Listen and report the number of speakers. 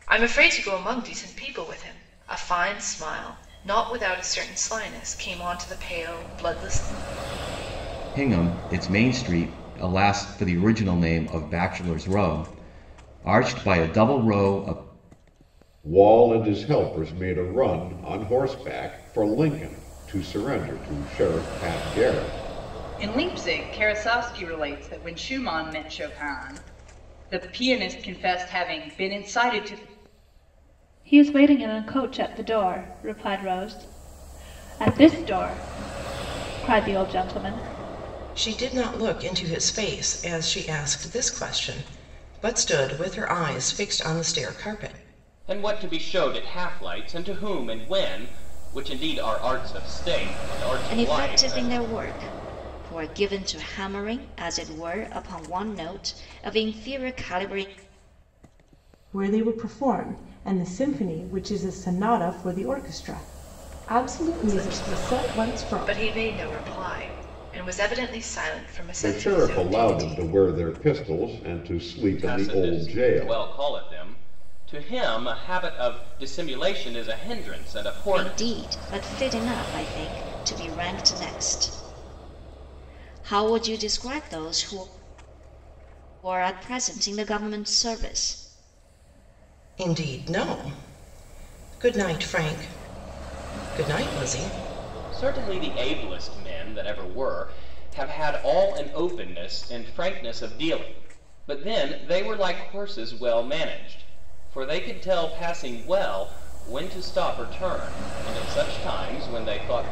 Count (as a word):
nine